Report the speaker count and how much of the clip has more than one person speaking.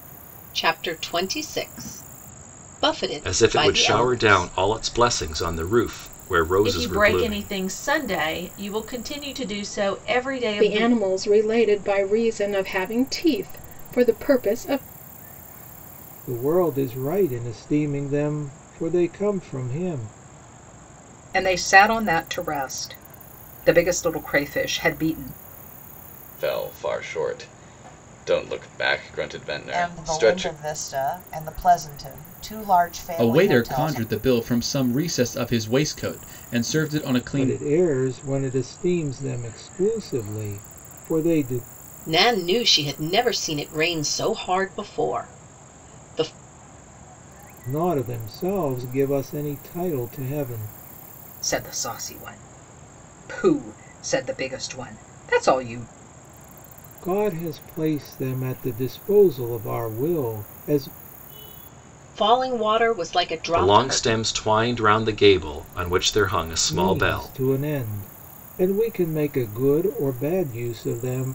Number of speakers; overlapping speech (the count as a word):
nine, about 9%